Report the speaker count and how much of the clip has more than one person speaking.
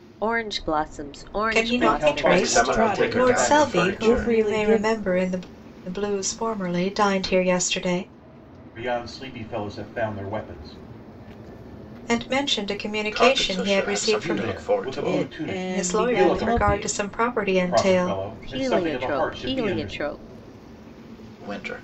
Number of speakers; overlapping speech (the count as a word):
five, about 44%